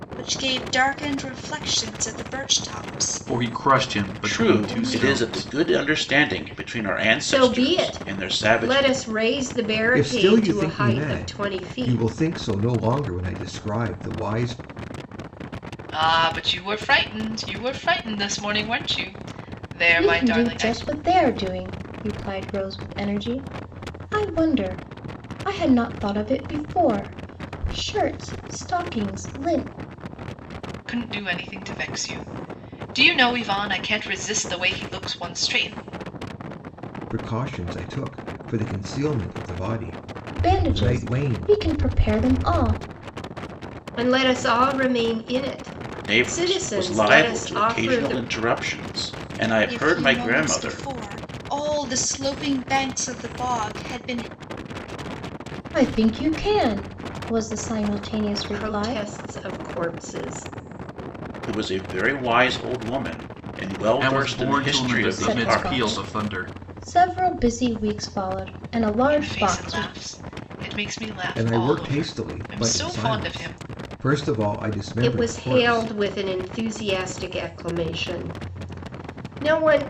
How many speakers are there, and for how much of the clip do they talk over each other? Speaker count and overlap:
7, about 24%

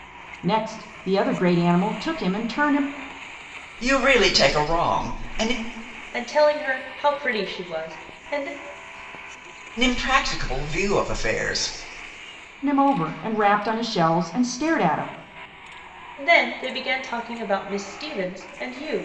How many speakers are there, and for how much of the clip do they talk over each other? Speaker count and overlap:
3, no overlap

